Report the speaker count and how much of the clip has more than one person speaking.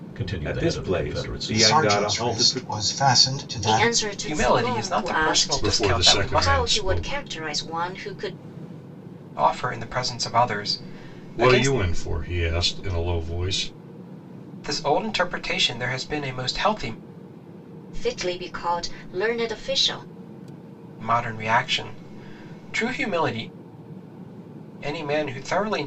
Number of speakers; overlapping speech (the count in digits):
6, about 24%